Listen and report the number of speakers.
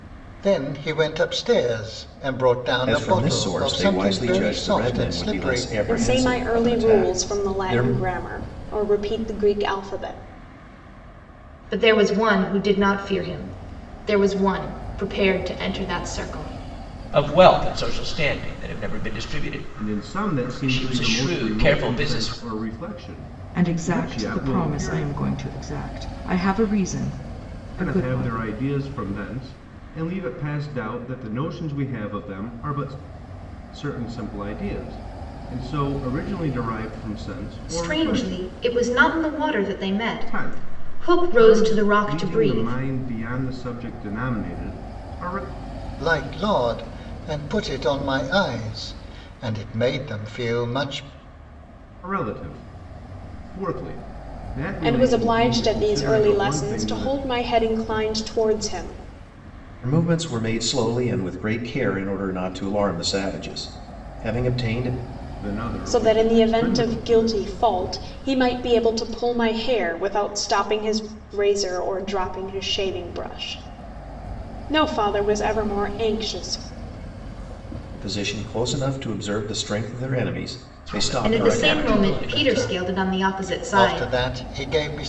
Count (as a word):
seven